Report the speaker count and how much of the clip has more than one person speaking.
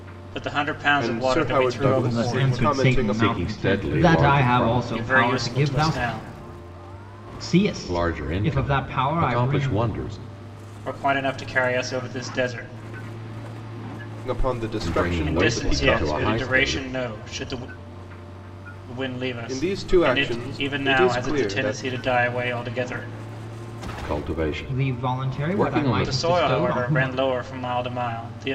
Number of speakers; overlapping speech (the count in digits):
4, about 49%